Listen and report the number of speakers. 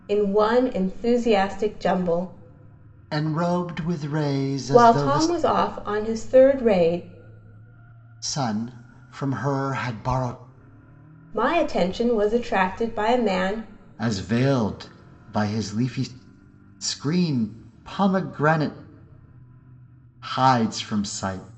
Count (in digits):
2